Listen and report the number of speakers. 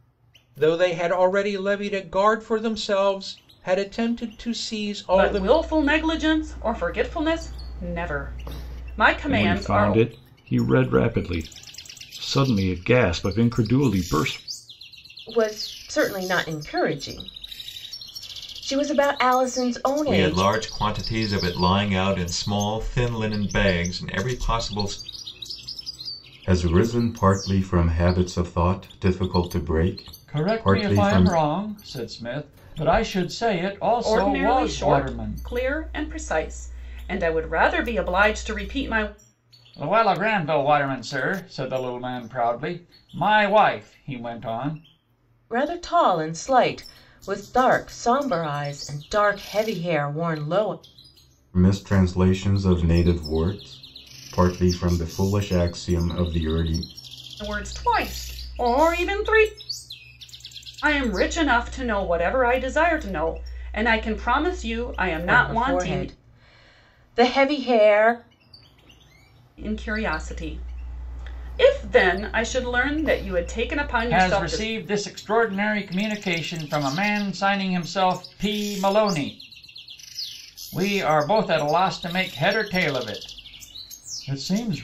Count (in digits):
7